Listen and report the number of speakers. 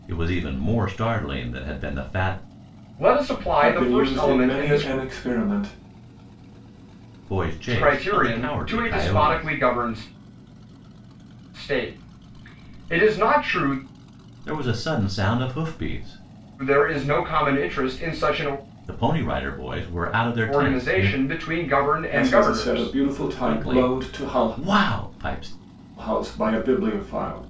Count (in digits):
3